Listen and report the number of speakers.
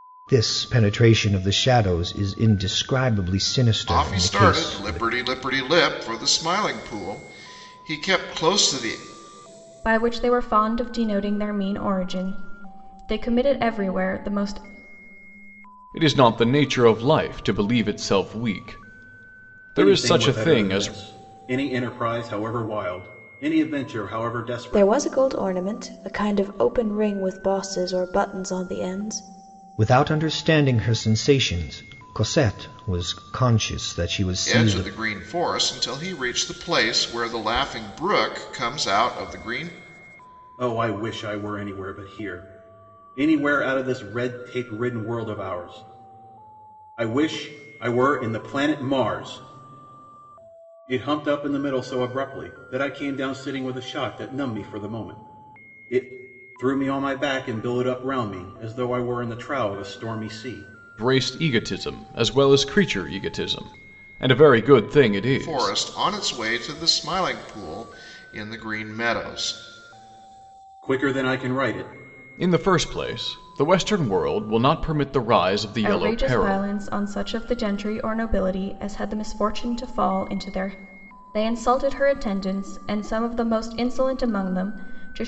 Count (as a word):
six